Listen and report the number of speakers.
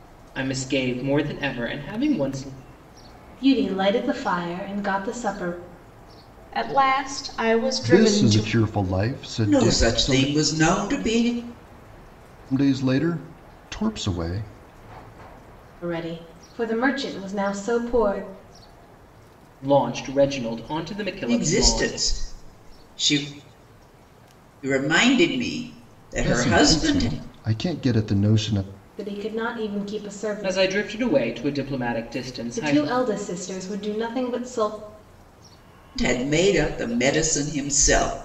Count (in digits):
5